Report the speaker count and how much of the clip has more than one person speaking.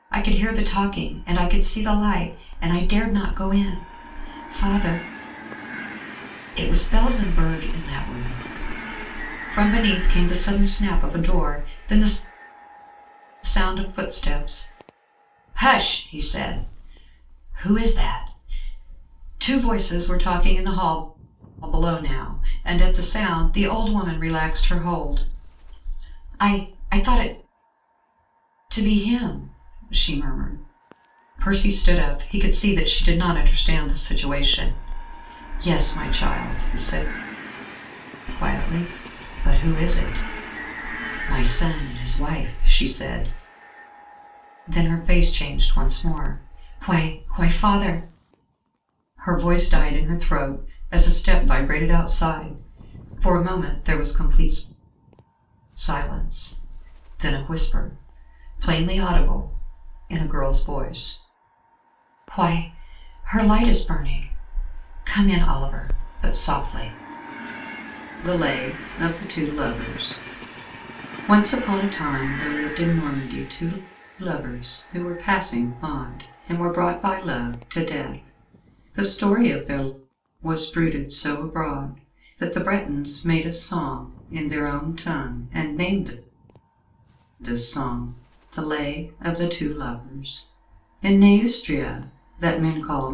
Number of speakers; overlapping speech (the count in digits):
1, no overlap